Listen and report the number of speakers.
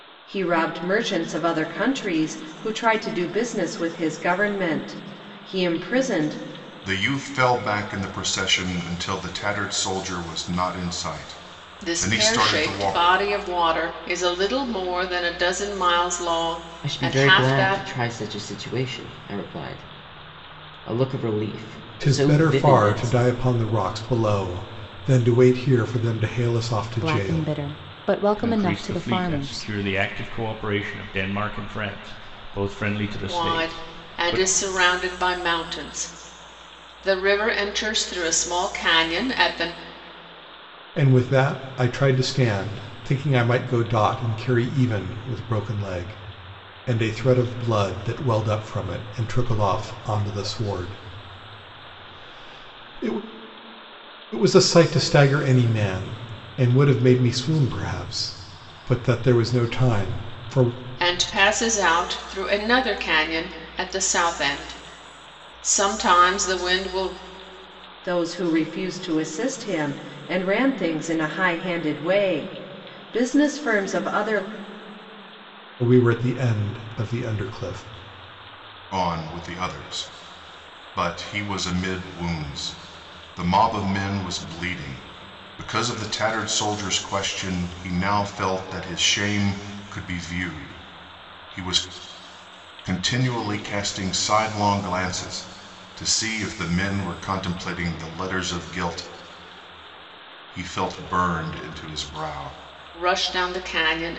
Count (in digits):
7